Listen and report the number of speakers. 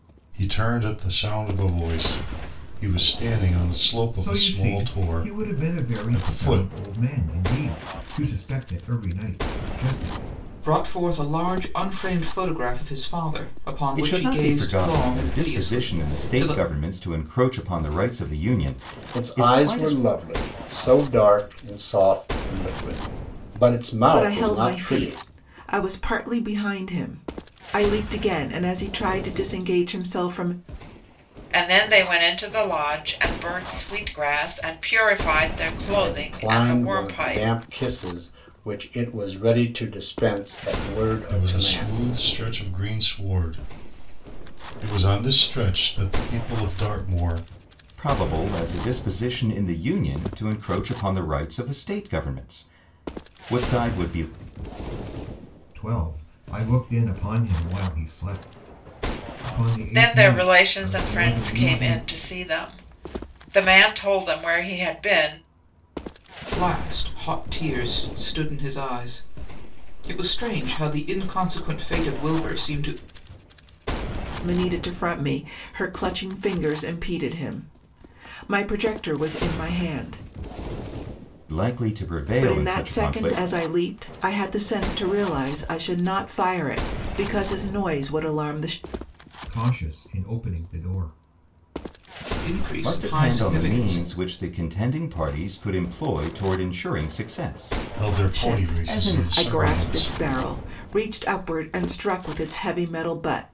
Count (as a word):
seven